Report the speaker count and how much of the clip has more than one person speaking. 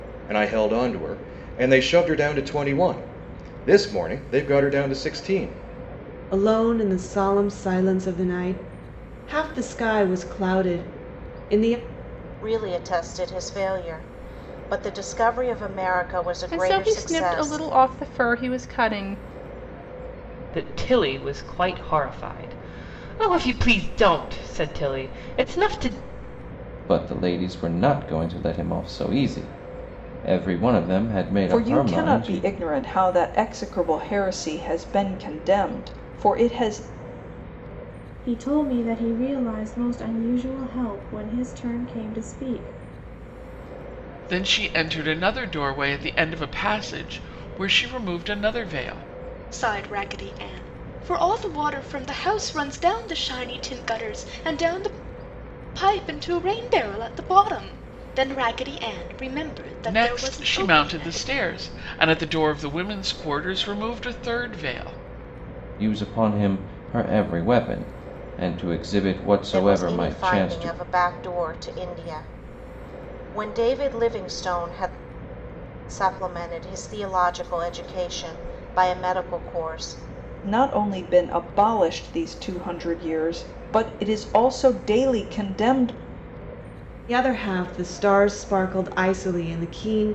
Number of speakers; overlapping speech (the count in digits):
10, about 6%